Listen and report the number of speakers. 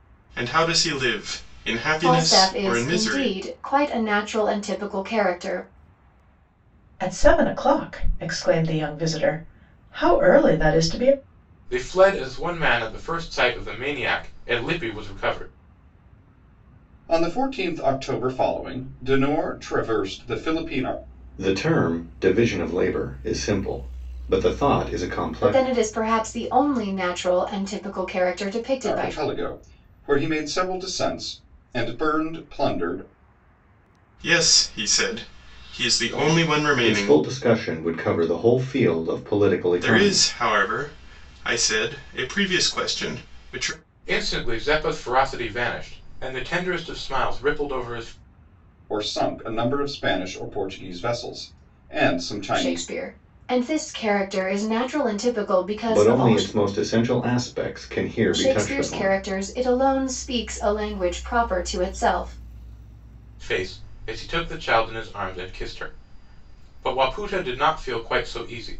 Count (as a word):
six